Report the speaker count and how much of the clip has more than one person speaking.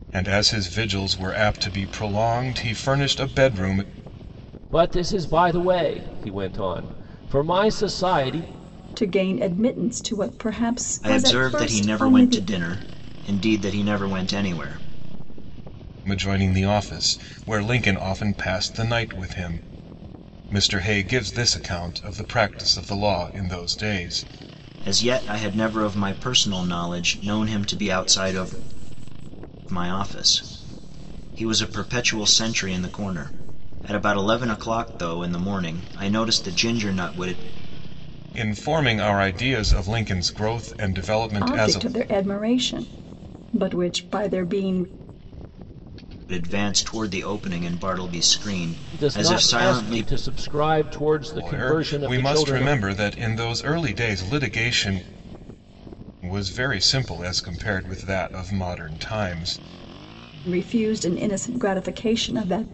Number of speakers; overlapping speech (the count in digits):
4, about 7%